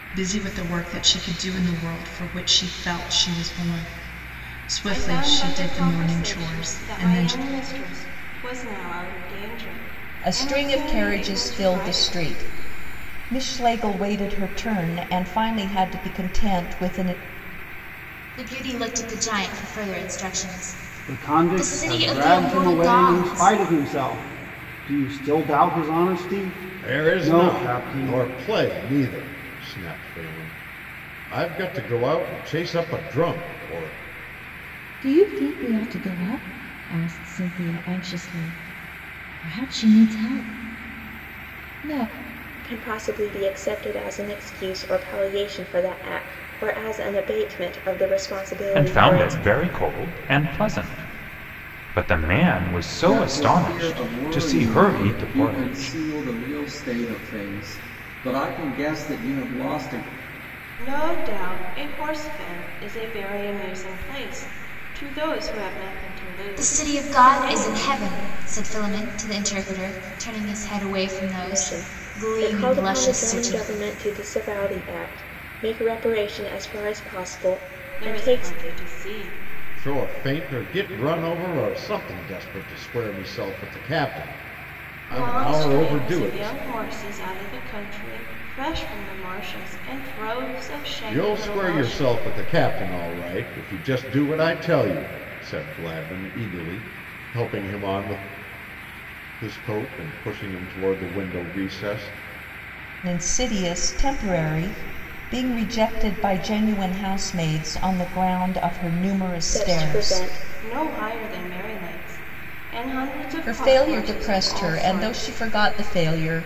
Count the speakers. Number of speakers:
ten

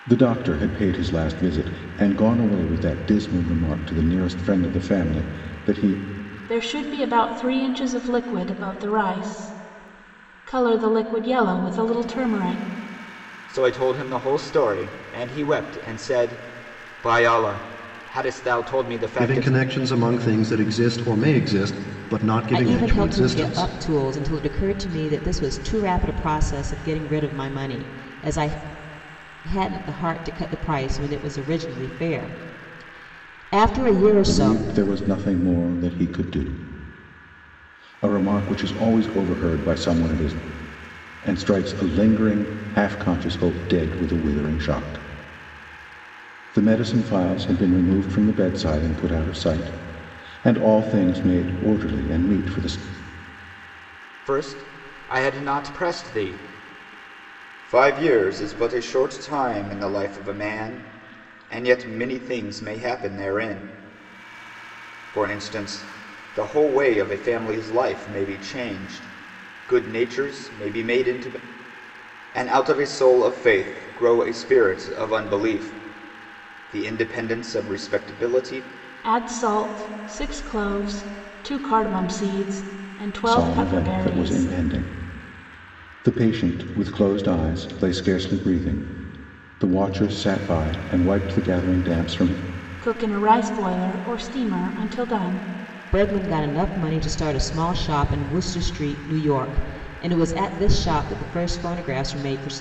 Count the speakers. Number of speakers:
five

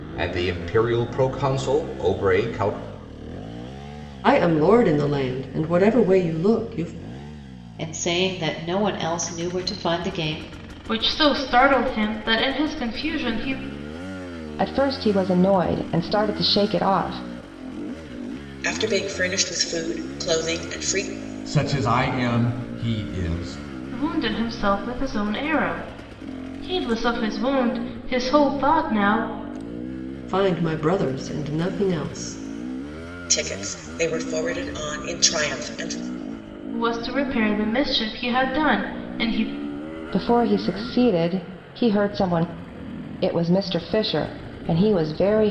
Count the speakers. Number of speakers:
seven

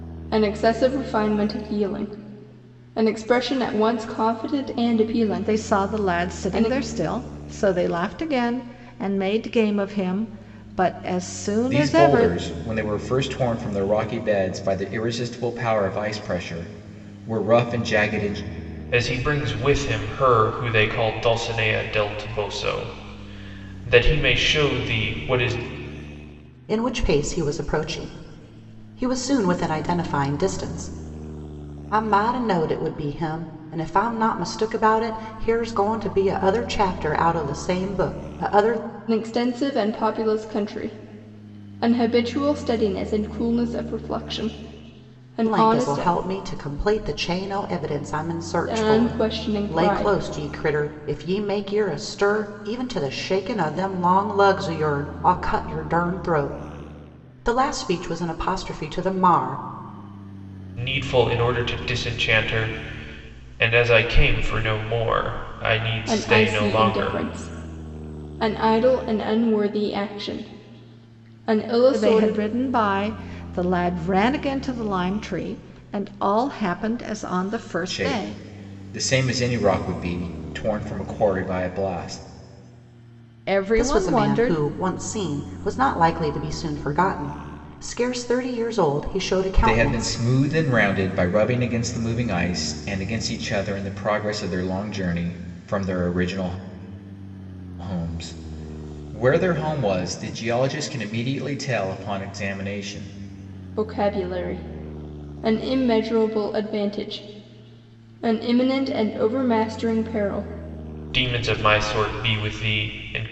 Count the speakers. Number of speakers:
five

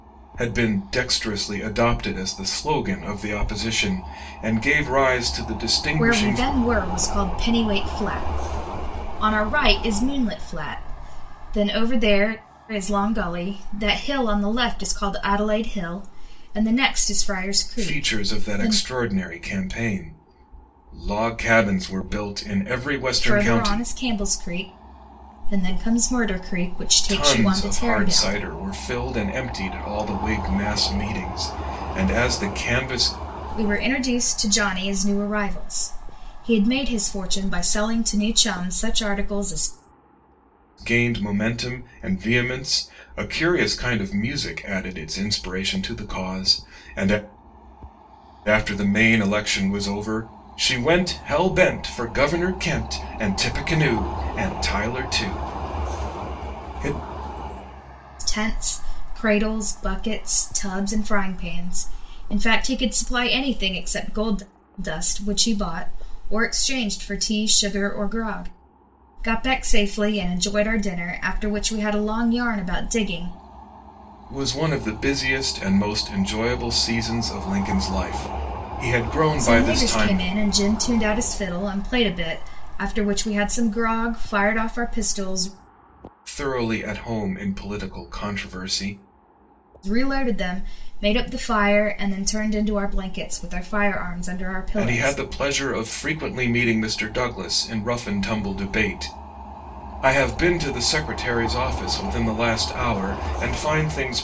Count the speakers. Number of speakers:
two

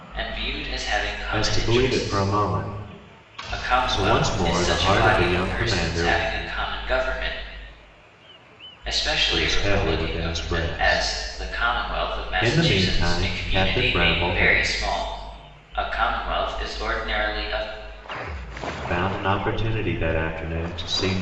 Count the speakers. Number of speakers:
two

